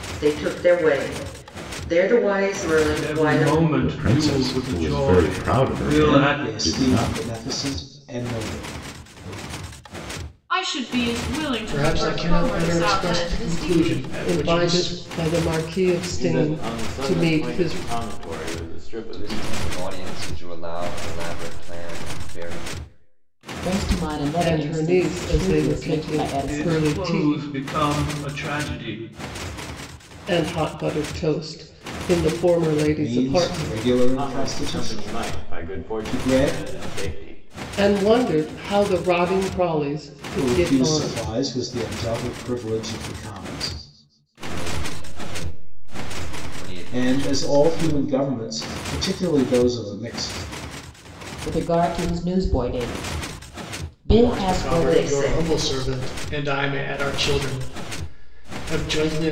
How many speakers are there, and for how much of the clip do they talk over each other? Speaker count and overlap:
10, about 33%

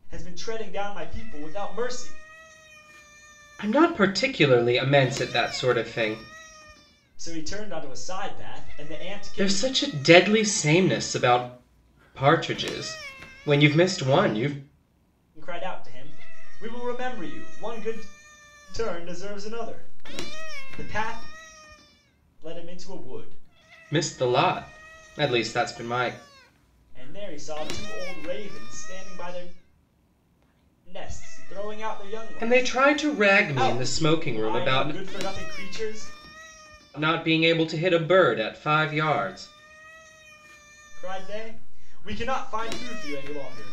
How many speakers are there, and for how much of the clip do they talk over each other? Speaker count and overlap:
2, about 5%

